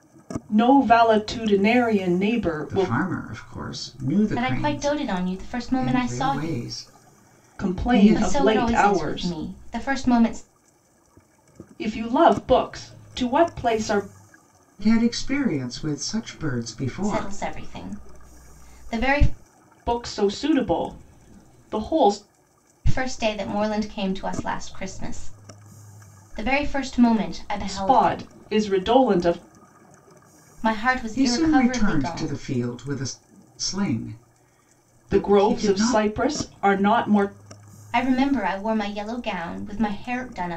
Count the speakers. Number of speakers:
three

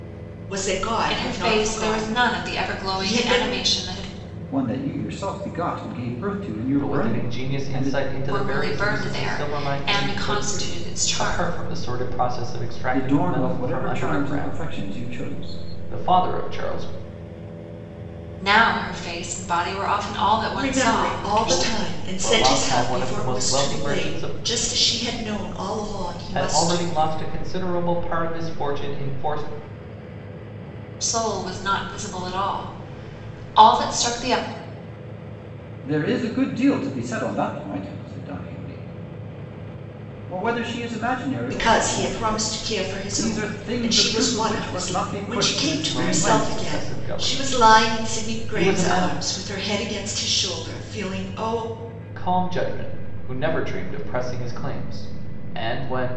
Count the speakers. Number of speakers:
four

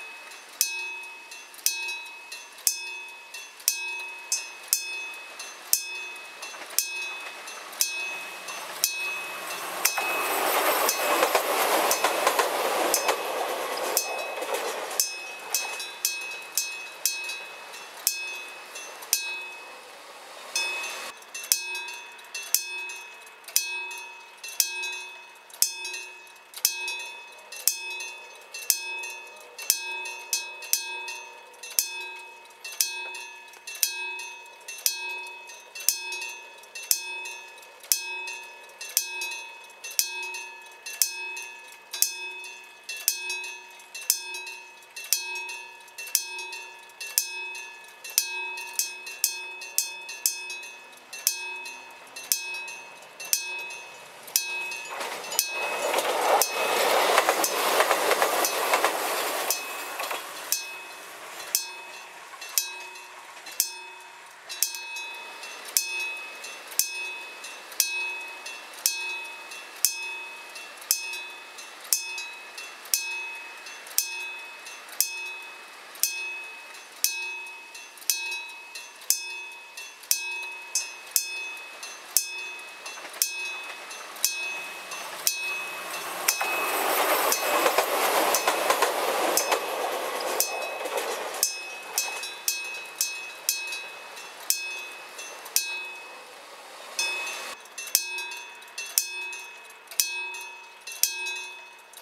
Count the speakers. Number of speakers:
zero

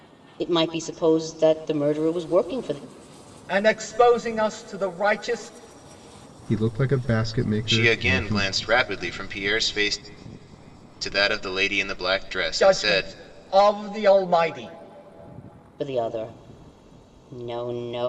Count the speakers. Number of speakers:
four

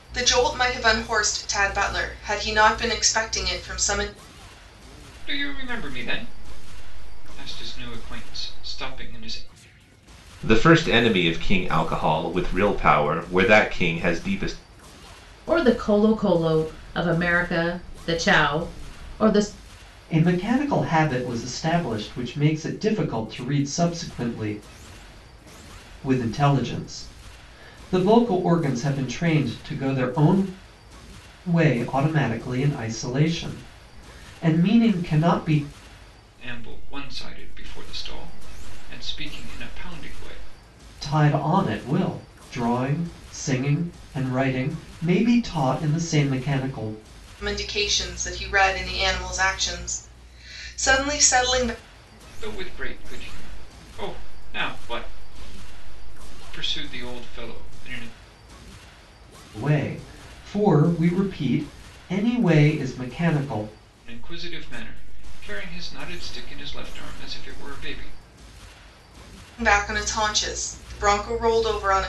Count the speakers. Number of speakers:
five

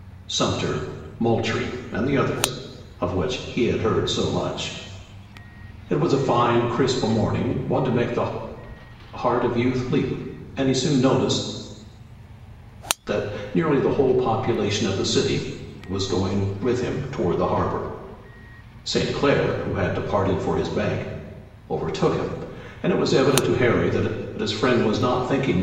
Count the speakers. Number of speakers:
one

